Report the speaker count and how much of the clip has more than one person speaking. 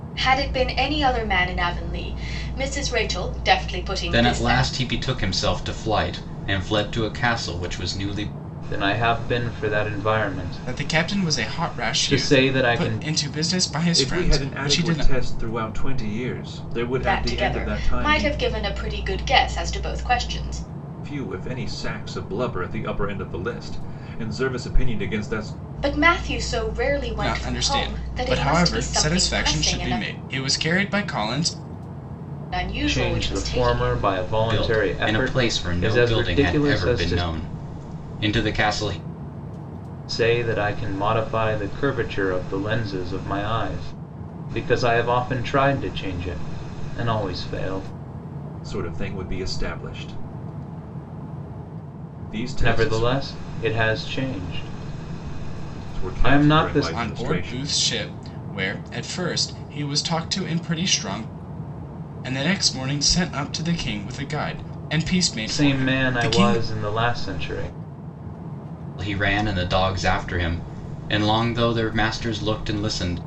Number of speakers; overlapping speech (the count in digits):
5, about 22%